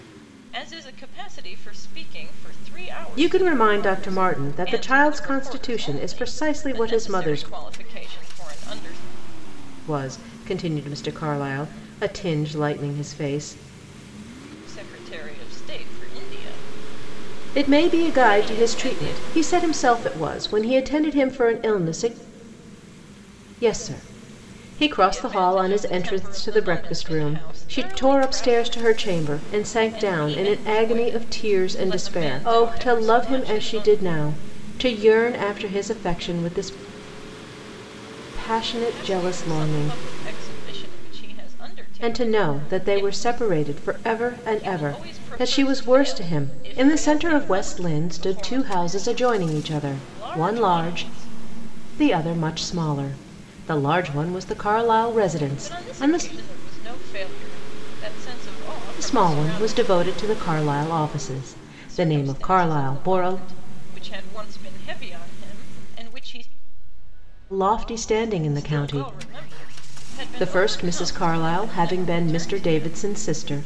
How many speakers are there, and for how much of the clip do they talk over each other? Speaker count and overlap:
2, about 37%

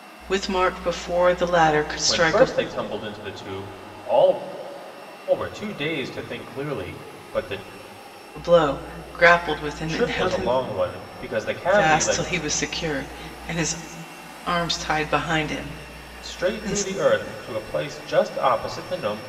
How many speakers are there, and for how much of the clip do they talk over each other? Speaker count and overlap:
2, about 13%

